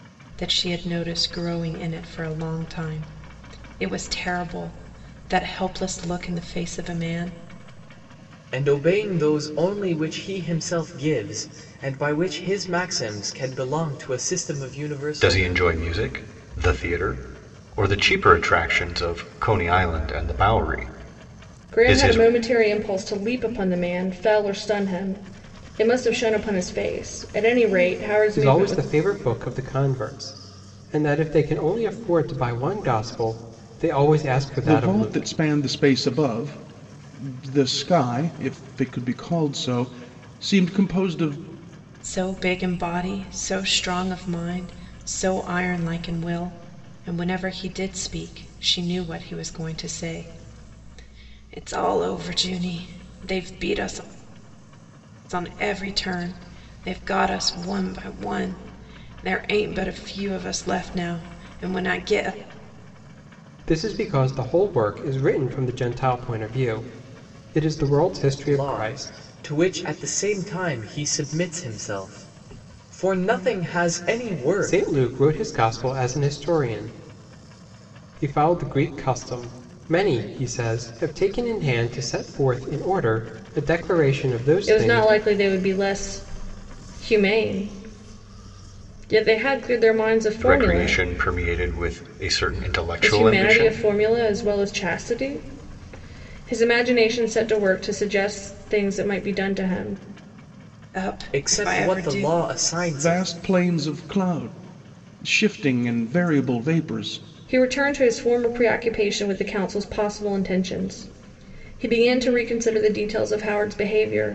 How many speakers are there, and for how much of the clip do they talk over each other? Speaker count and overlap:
6, about 6%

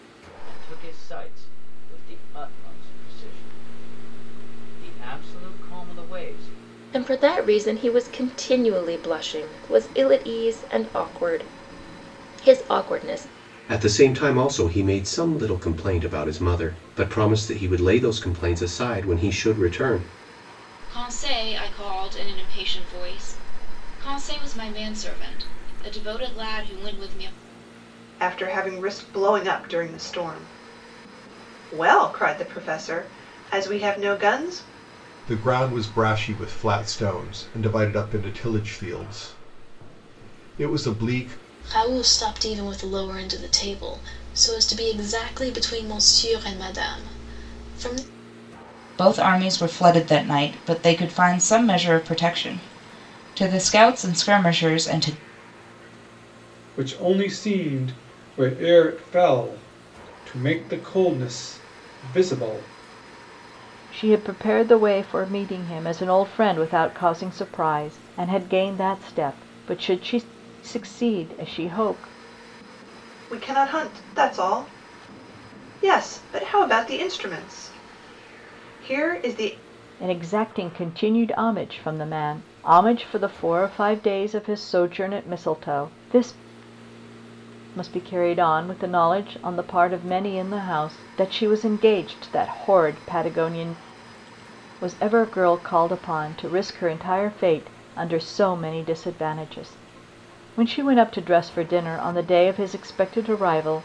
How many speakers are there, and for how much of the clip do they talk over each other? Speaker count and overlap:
10, no overlap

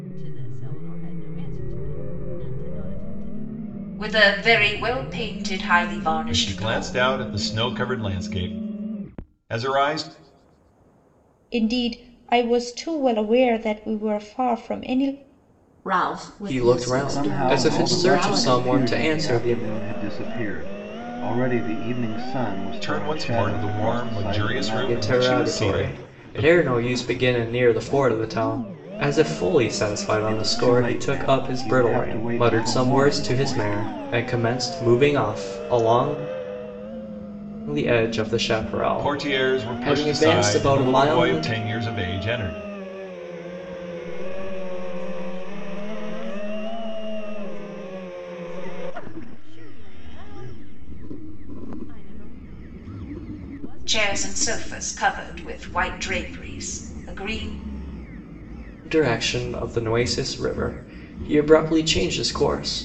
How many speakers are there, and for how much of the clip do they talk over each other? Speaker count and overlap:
7, about 24%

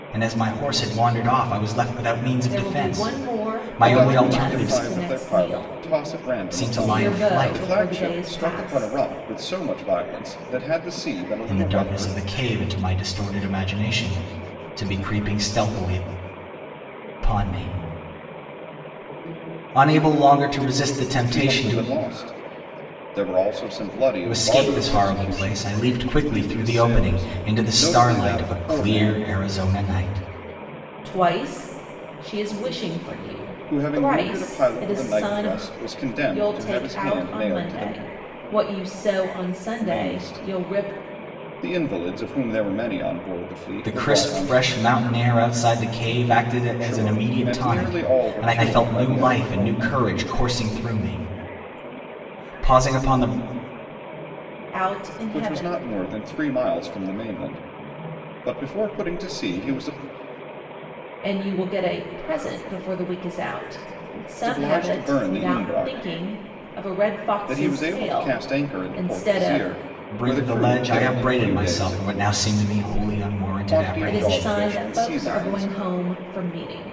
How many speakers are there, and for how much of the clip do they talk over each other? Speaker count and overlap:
3, about 38%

